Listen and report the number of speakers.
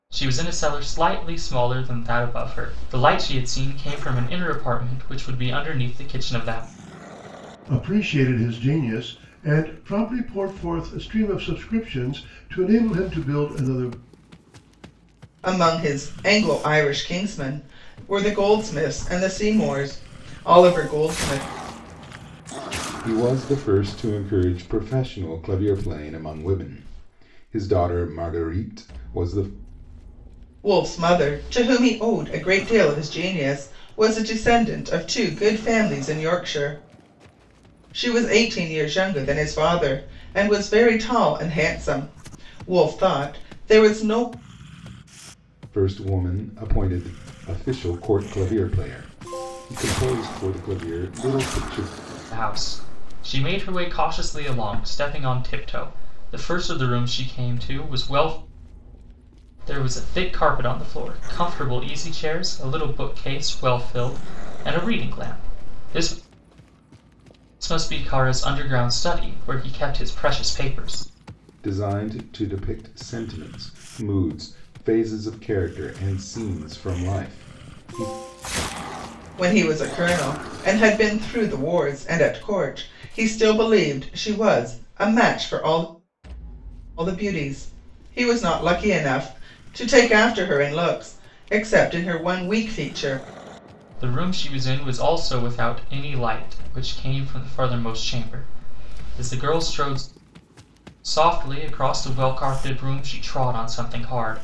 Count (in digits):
4